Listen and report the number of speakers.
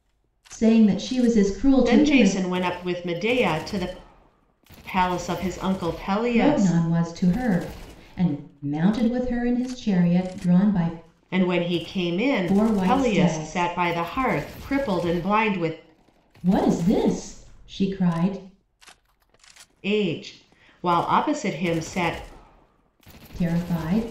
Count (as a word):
two